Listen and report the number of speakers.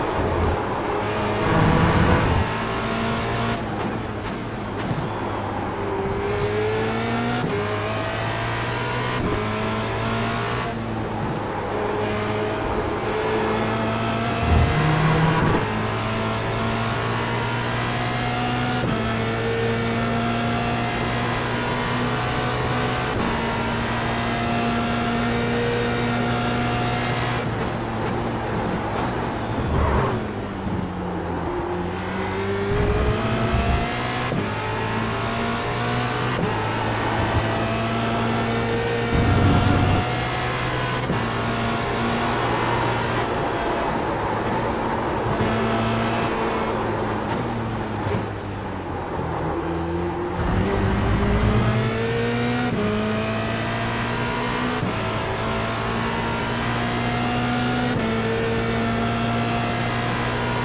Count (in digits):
0